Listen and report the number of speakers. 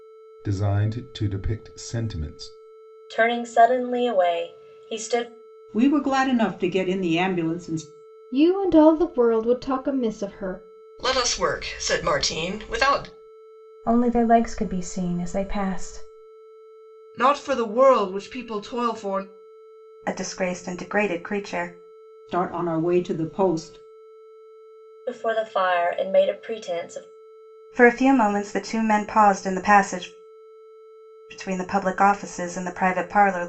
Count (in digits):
8